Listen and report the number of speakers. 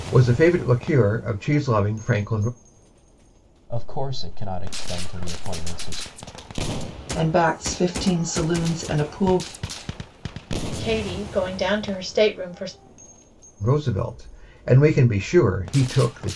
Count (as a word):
four